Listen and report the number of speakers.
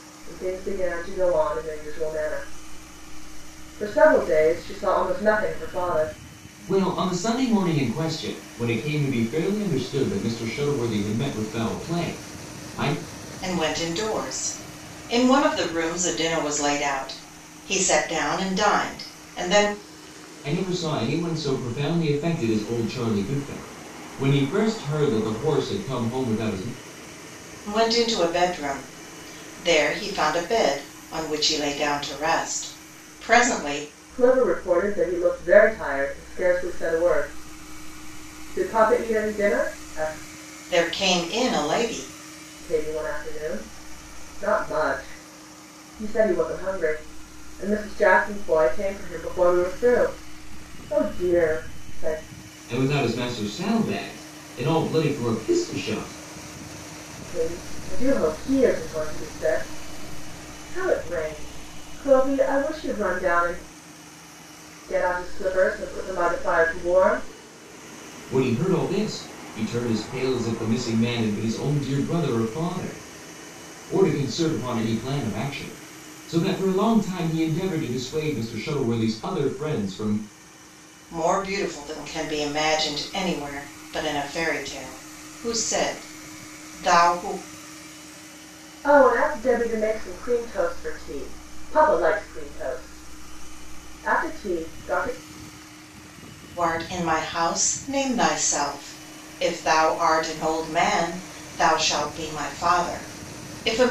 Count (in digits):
3